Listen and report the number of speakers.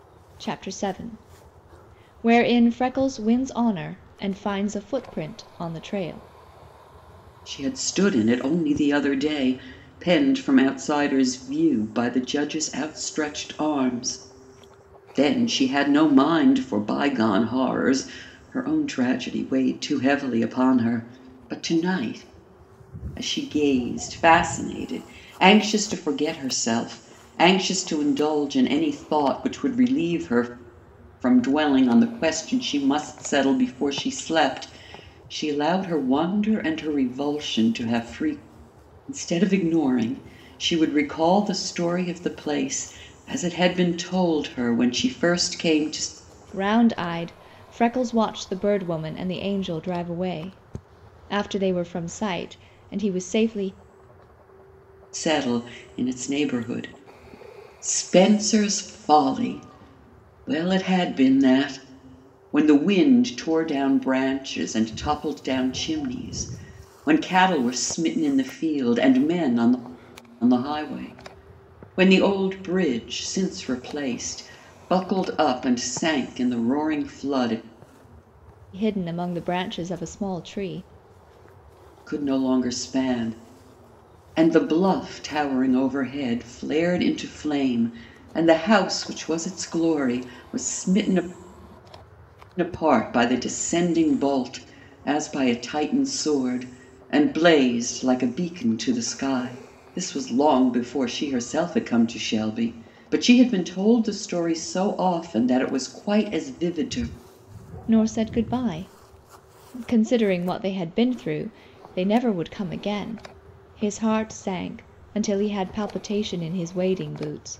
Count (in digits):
2